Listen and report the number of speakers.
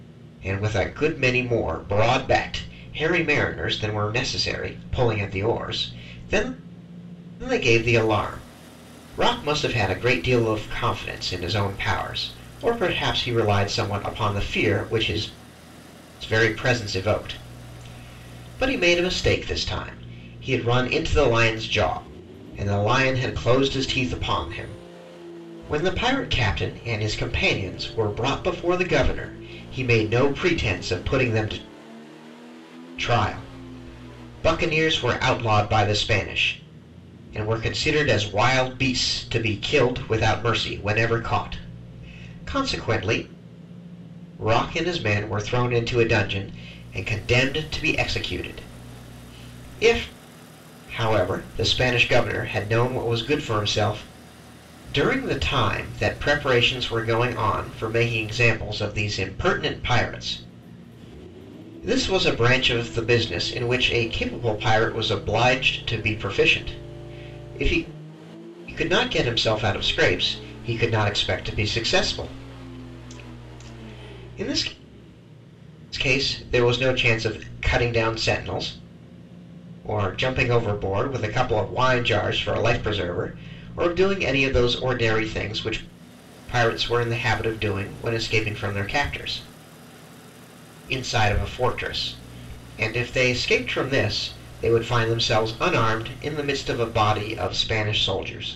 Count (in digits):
1